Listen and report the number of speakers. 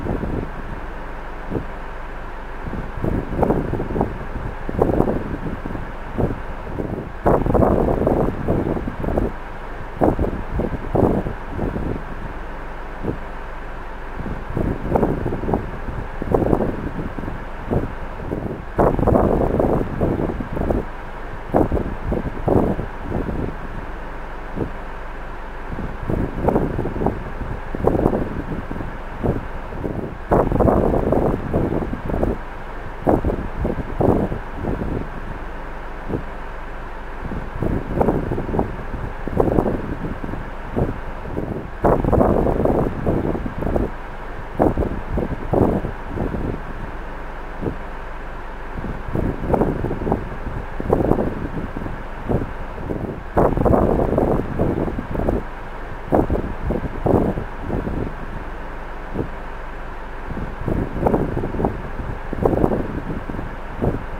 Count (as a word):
zero